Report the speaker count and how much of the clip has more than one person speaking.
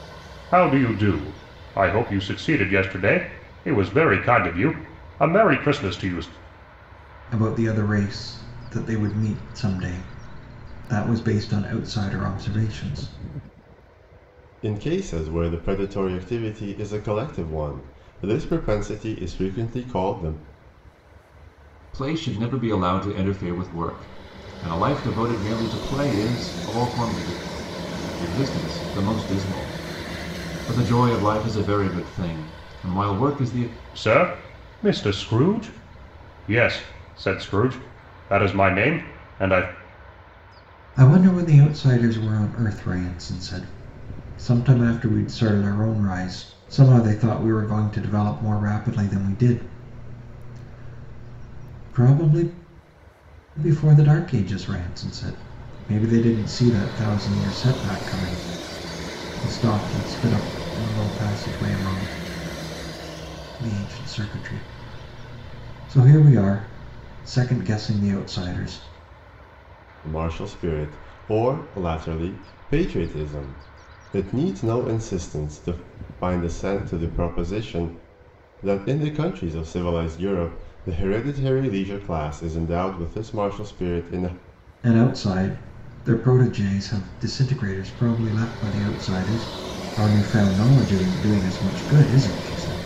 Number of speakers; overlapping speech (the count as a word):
four, no overlap